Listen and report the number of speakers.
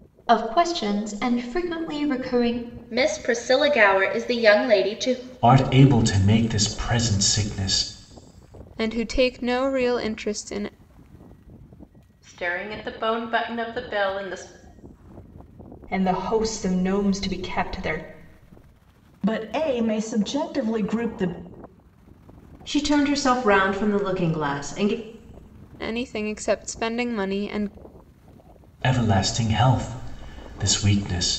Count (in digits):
8